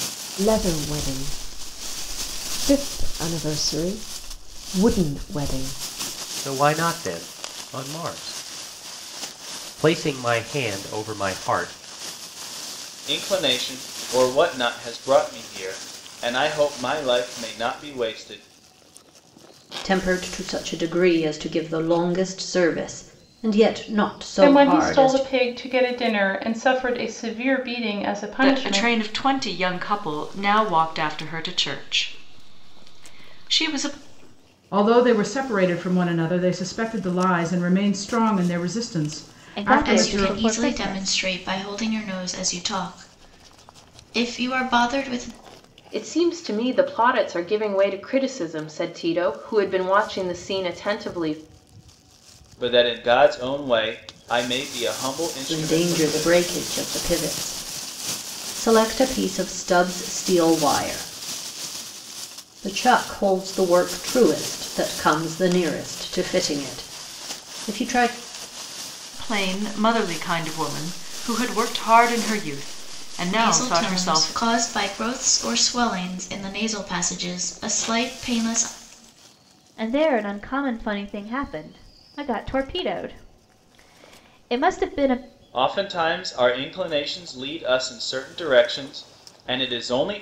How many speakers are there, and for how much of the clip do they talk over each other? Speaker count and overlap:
ten, about 6%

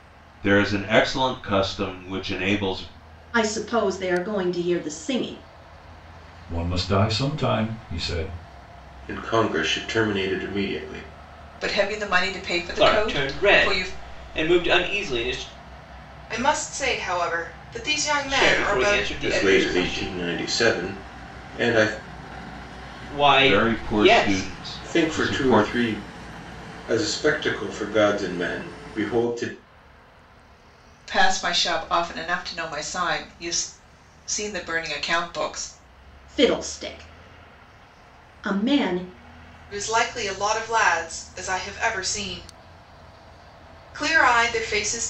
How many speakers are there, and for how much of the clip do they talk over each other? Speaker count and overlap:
seven, about 11%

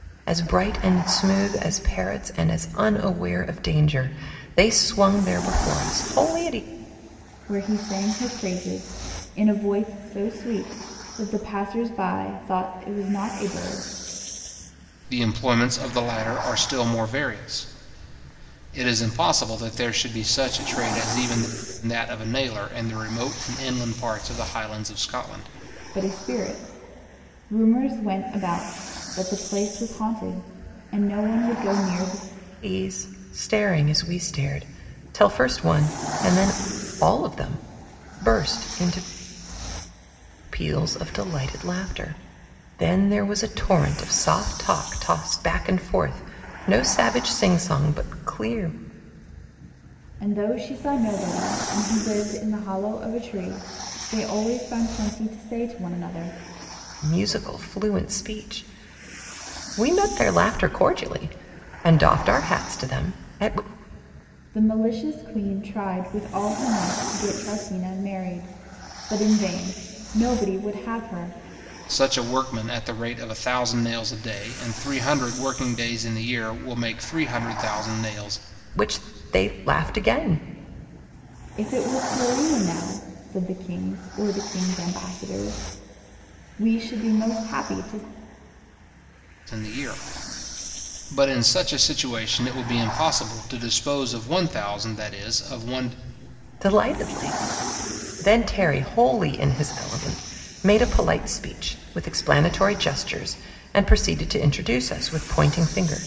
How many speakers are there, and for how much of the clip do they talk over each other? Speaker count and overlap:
three, no overlap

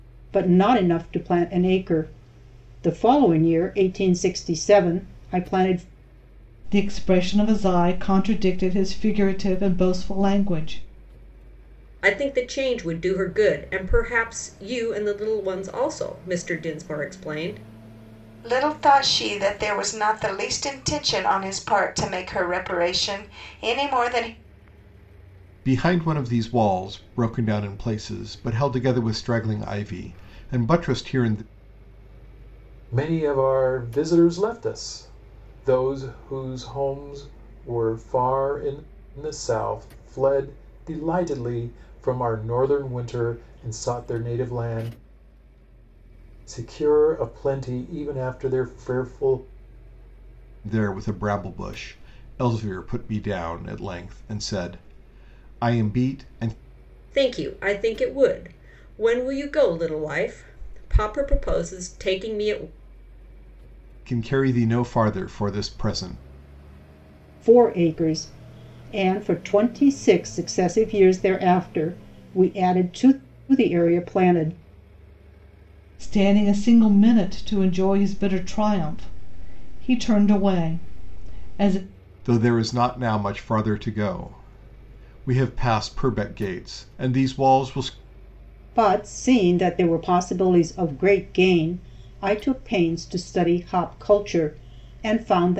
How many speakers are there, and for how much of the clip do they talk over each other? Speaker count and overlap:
six, no overlap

